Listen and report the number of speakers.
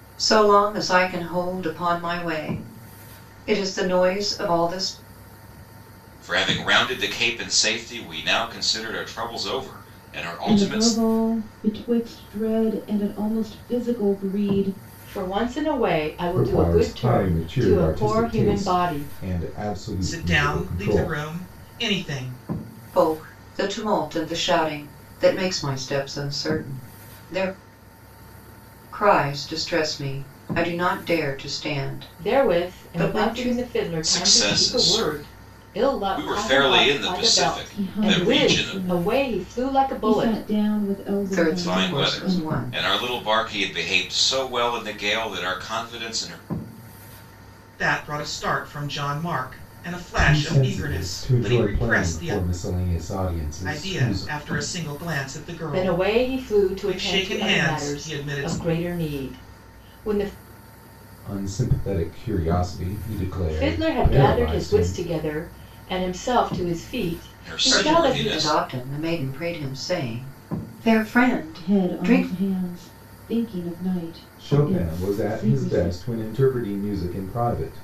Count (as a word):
six